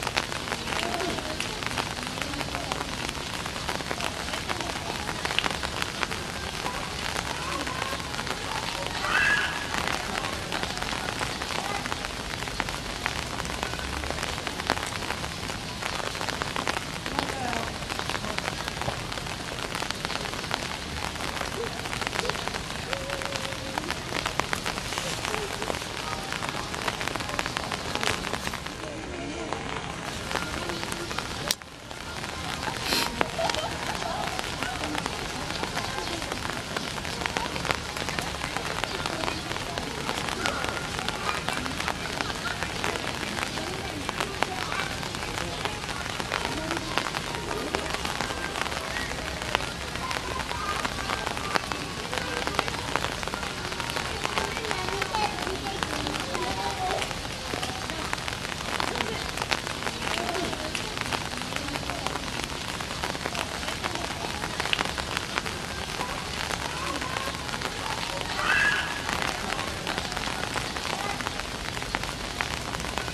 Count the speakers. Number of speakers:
0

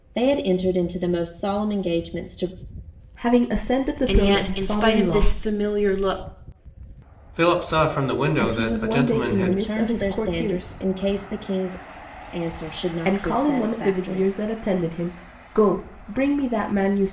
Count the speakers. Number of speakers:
4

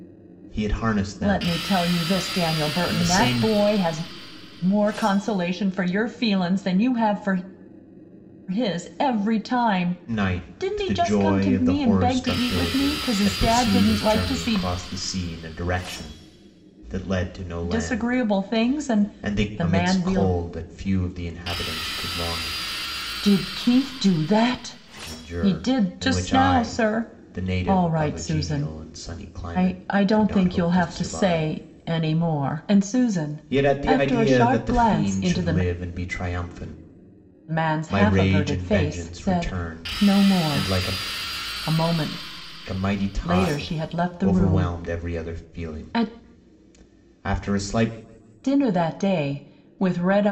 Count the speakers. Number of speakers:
2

